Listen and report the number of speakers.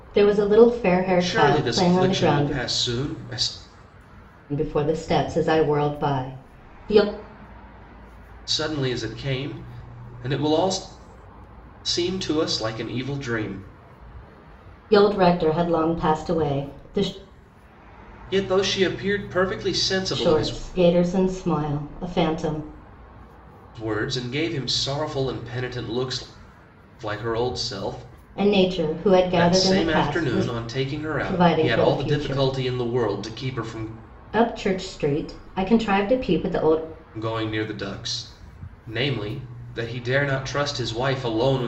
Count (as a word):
two